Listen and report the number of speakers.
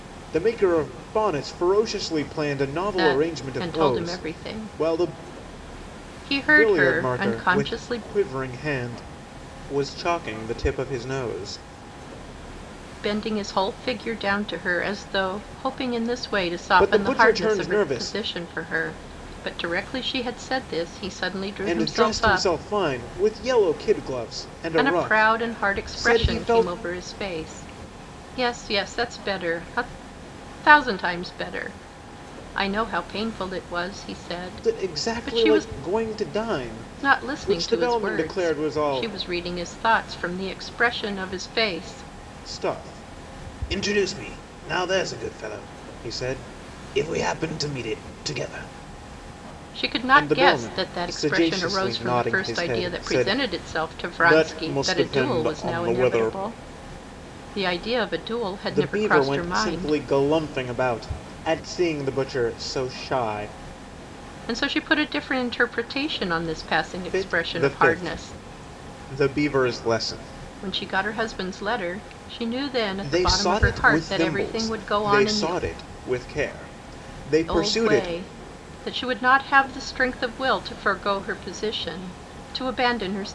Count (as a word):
two